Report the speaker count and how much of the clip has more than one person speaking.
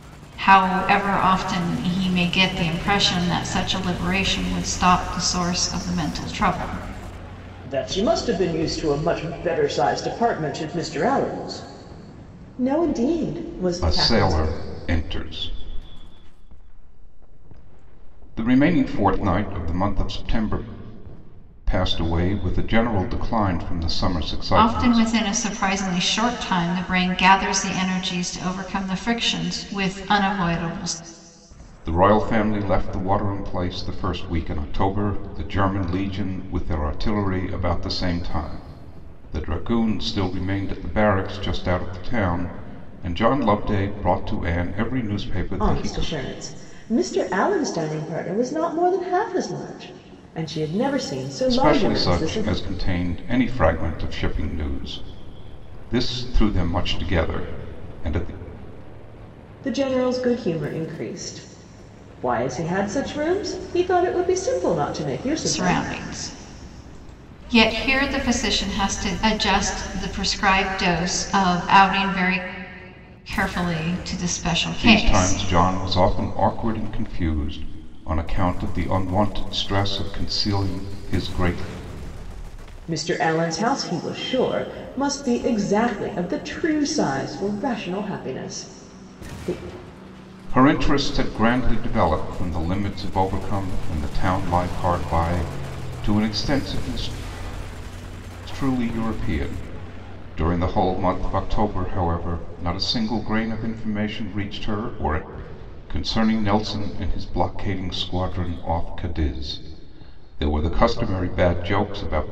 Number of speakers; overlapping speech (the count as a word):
three, about 4%